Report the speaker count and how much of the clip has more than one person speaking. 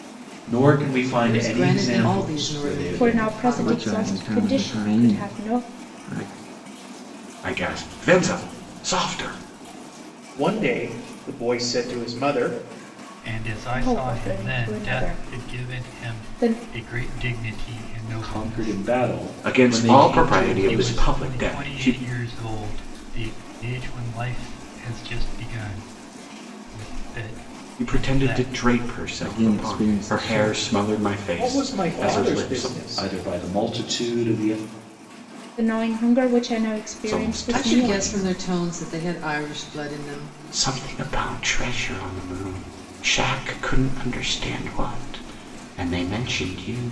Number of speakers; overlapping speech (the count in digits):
7, about 34%